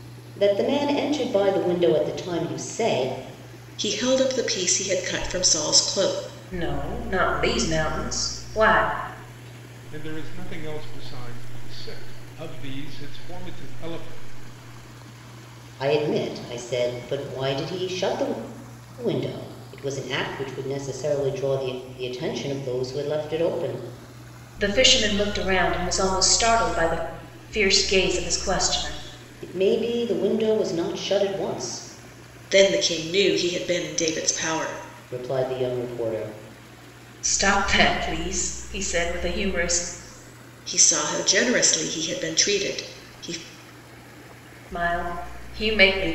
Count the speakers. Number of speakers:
4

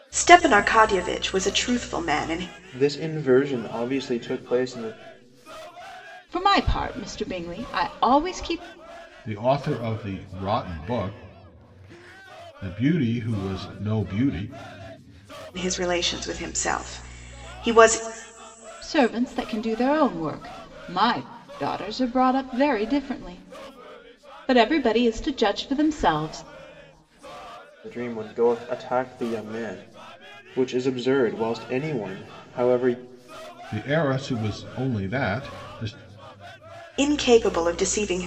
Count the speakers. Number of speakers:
4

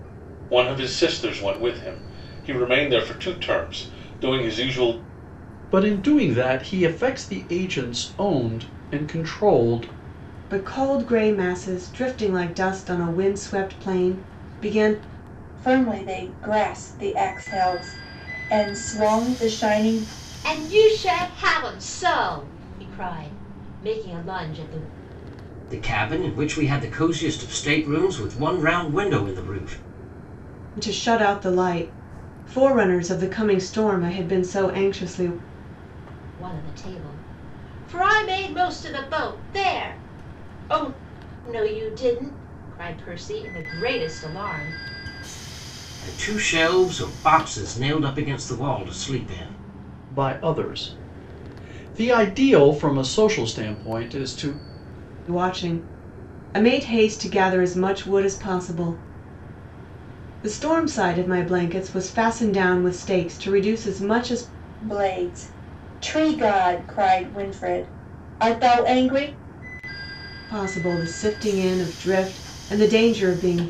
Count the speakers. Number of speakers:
6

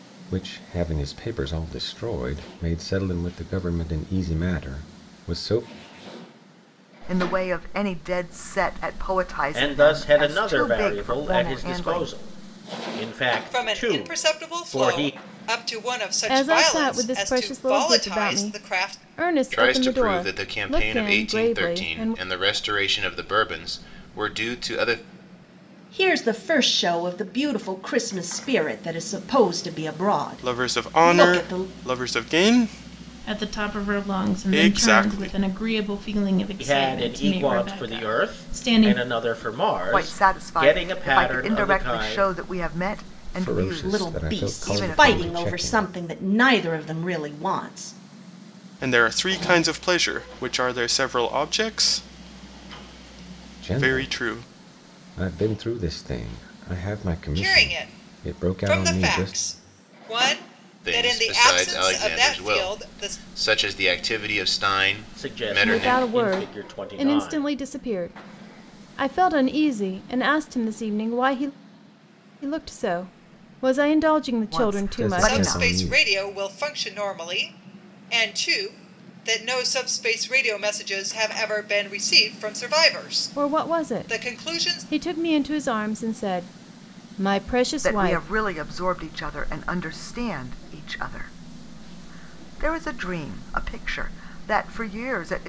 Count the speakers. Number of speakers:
9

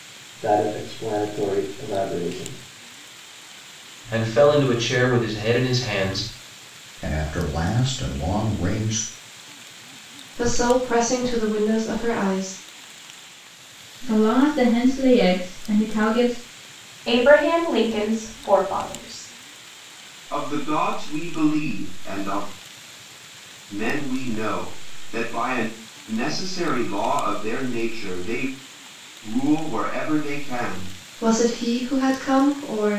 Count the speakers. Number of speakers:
7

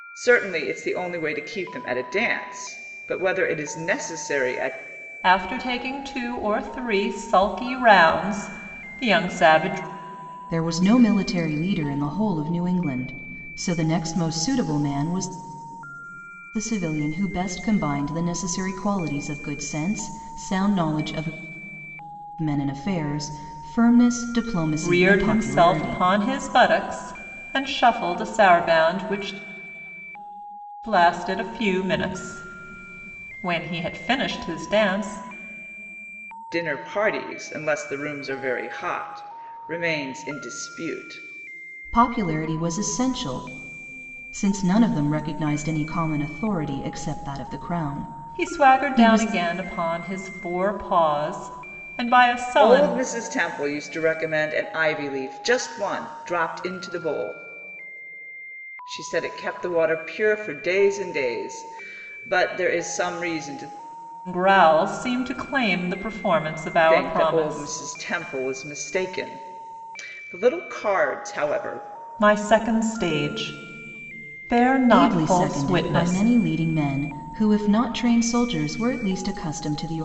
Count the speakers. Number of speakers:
3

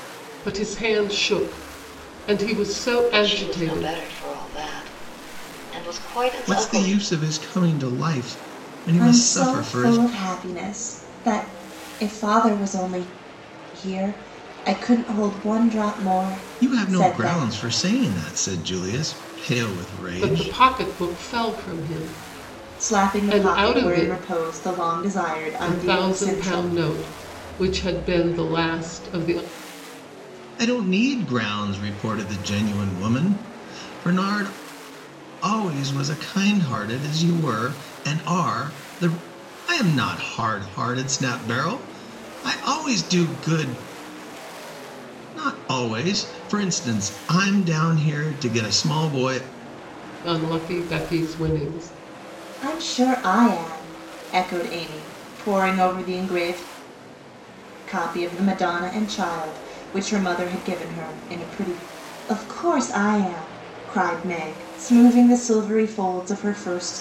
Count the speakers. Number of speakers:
4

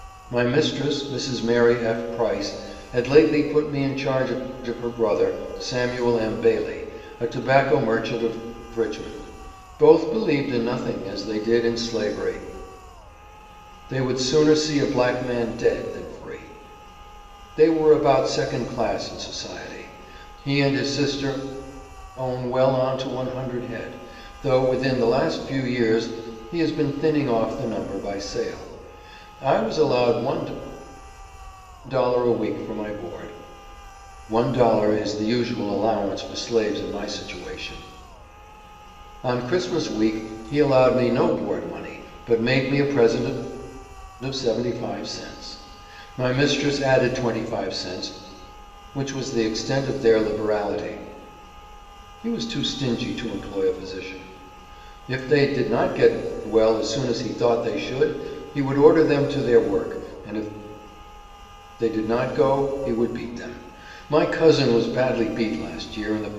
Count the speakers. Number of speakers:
1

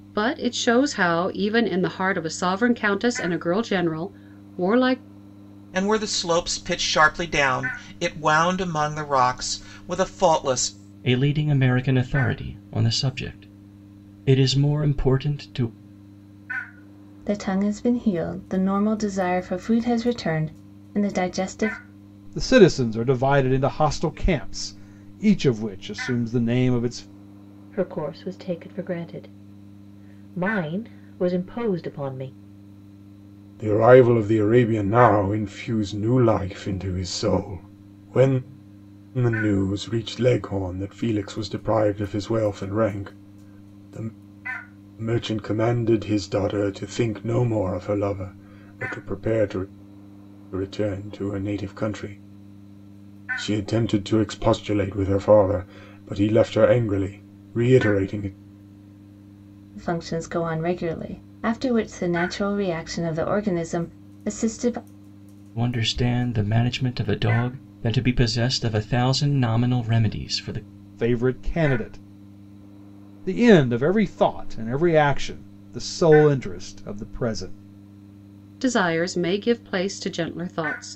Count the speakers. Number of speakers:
7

